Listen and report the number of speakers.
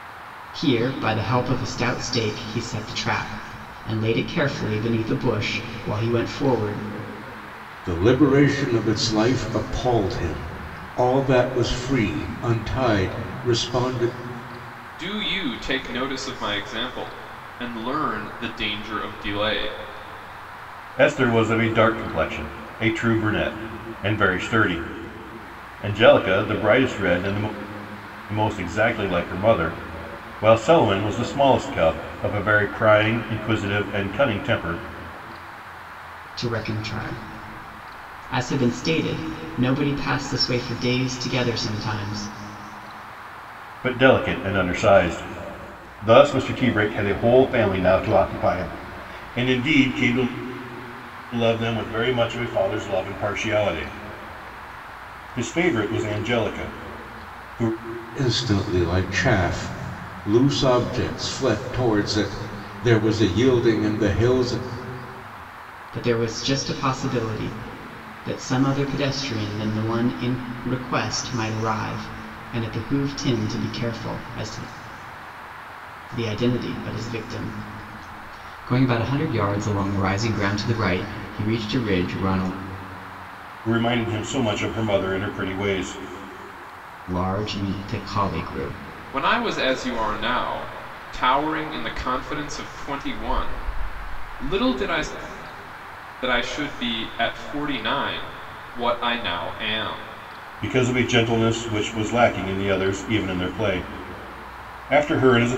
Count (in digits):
4